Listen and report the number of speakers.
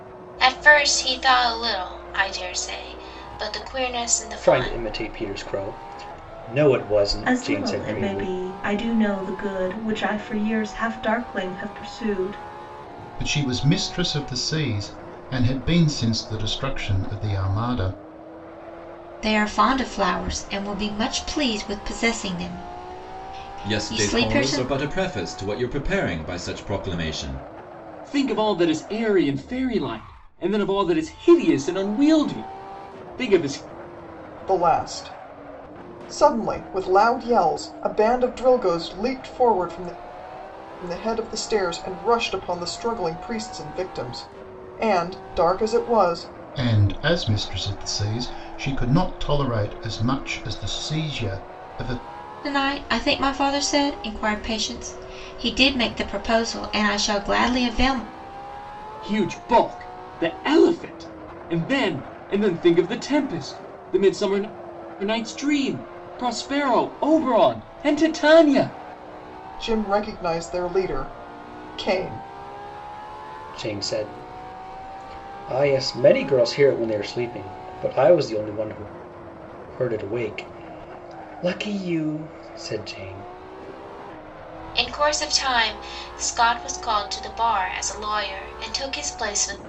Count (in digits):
8